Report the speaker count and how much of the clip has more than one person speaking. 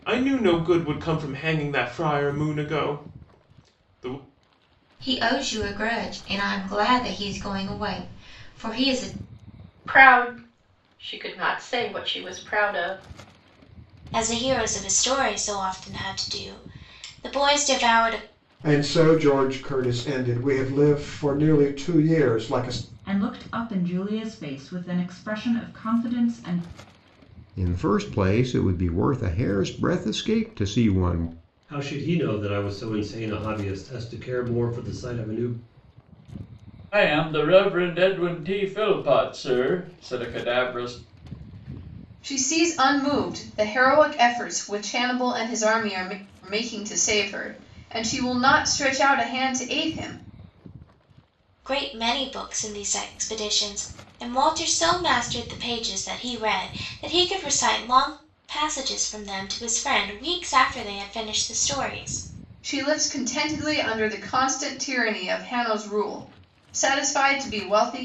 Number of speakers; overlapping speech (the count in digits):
10, no overlap